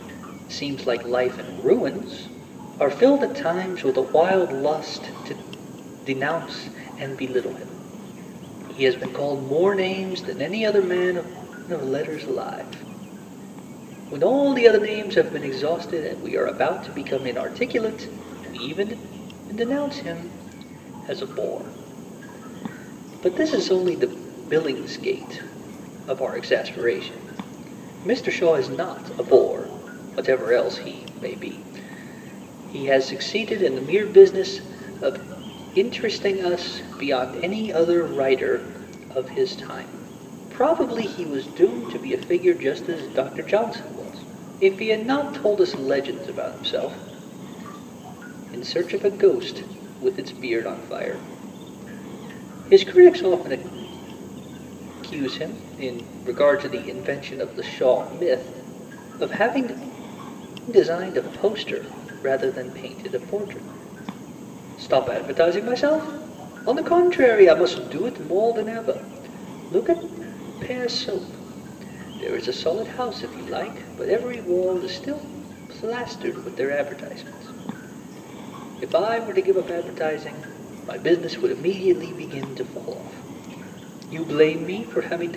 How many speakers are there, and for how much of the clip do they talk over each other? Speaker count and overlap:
1, no overlap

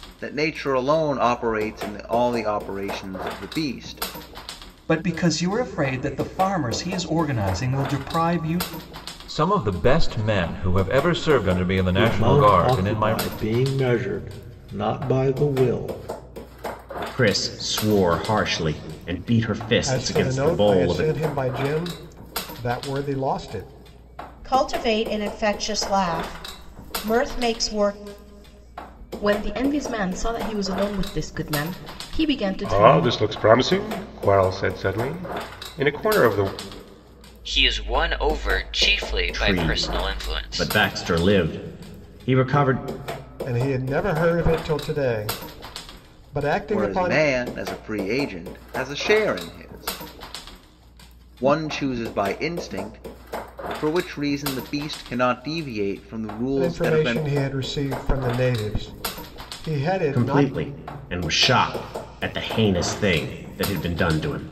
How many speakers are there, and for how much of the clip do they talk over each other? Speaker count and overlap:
10, about 10%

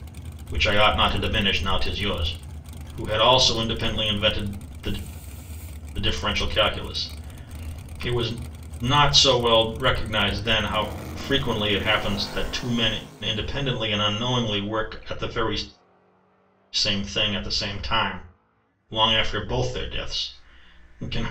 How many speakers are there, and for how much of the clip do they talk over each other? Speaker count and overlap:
1, no overlap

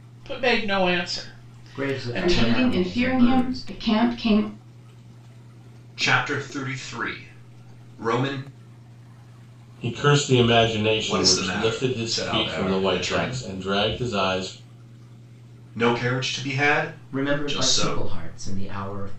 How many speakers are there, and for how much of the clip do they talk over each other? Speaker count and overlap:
5, about 28%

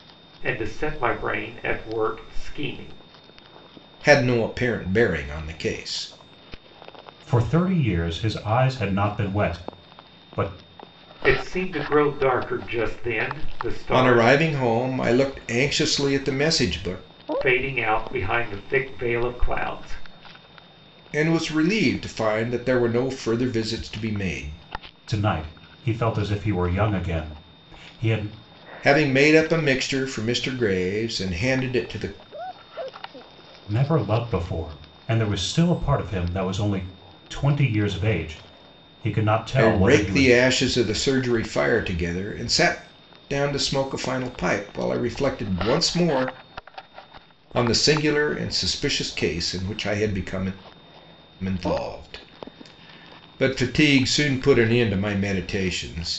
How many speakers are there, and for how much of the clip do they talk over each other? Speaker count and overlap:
3, about 2%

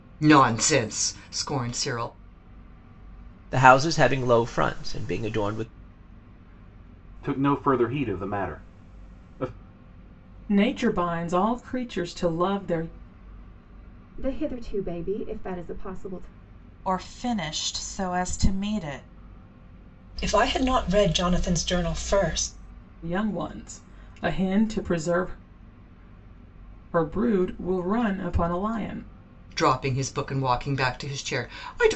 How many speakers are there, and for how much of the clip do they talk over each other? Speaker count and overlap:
7, no overlap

